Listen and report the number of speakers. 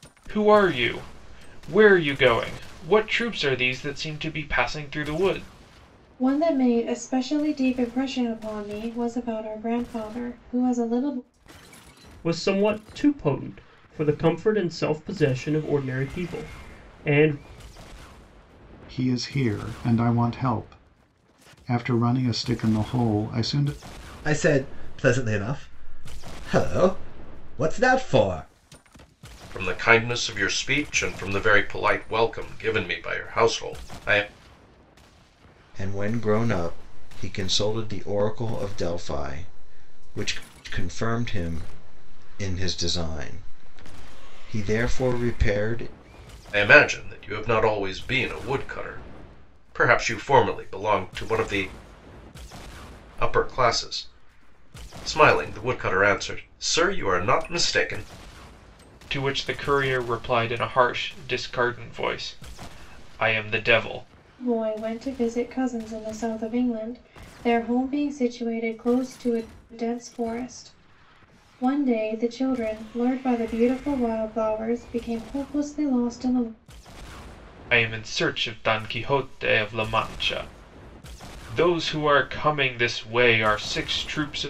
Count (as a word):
seven